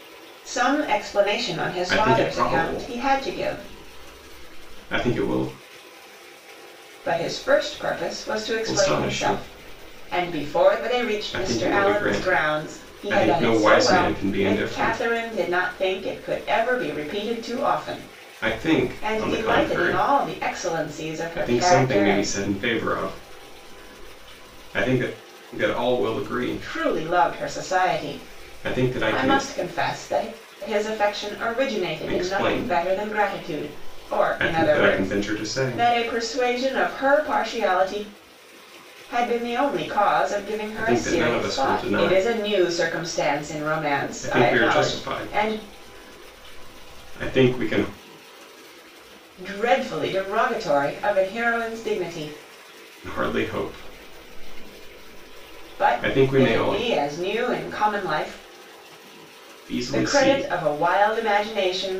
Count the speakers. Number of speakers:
2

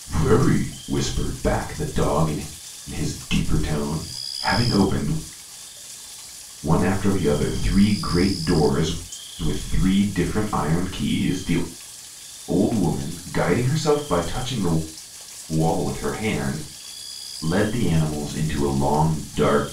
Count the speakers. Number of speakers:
1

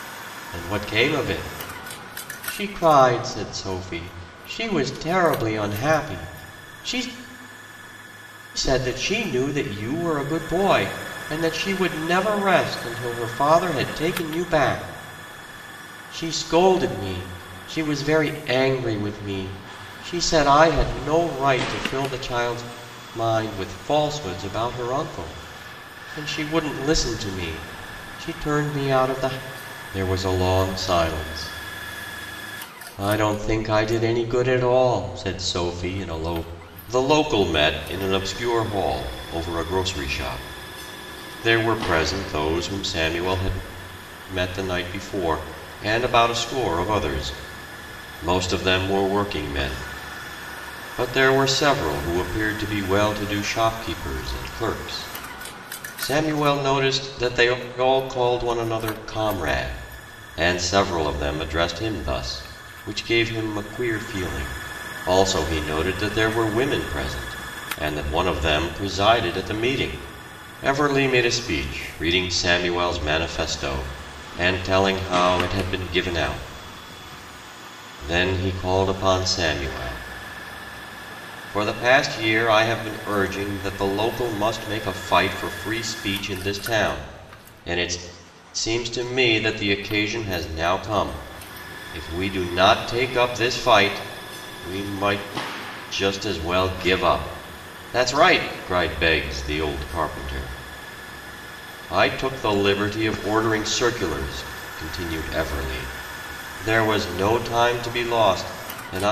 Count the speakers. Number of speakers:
1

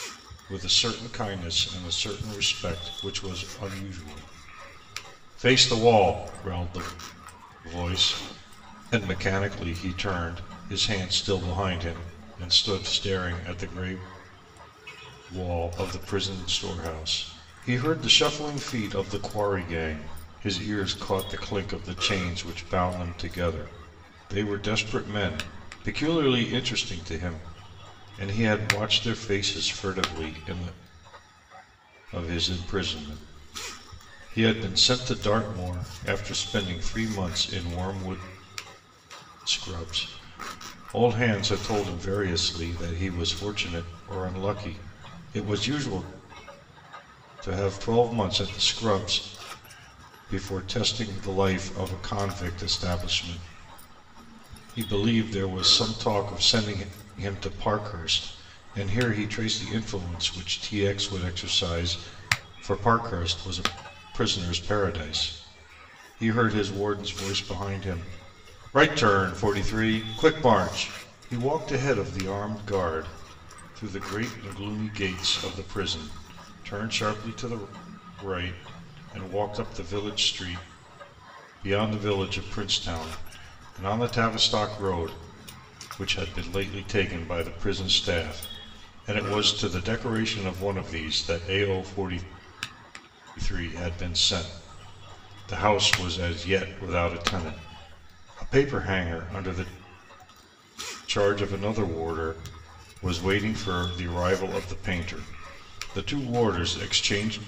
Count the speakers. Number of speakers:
1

